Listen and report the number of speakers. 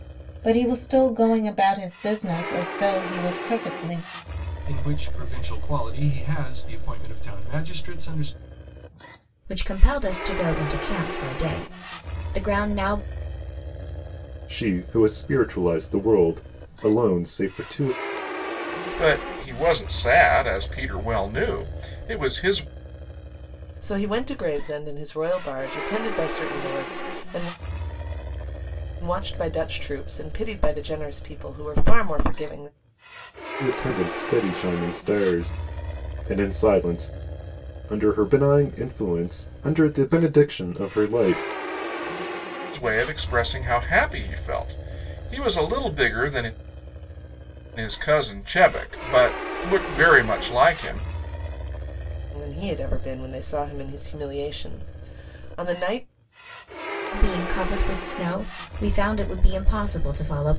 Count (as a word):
six